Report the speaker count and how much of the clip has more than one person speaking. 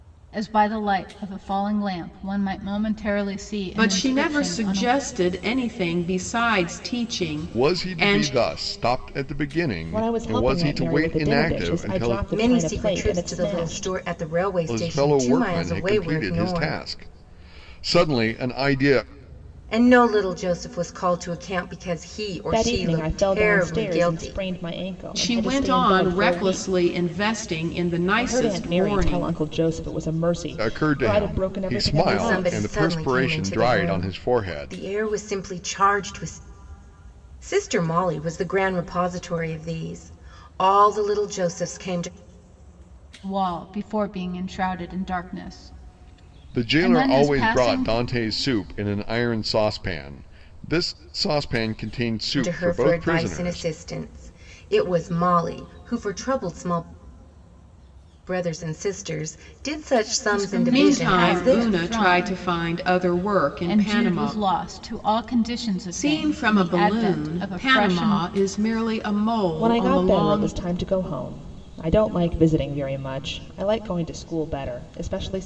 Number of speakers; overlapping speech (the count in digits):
5, about 35%